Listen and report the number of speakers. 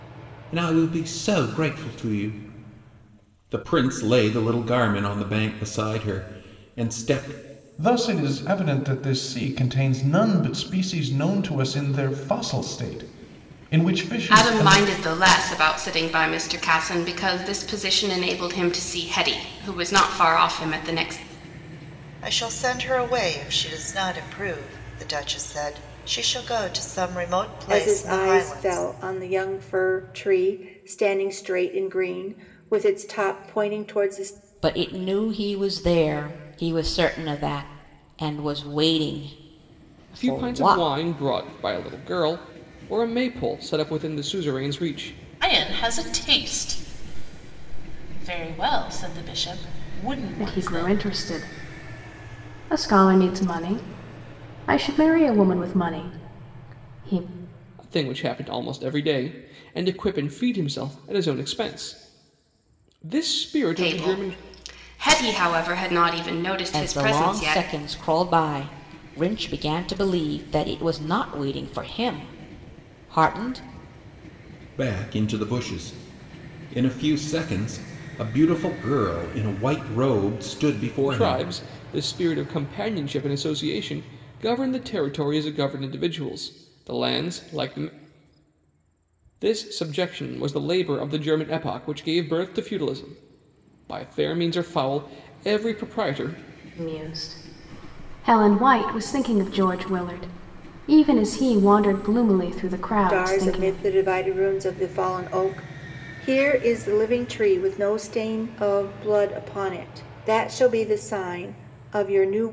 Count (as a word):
nine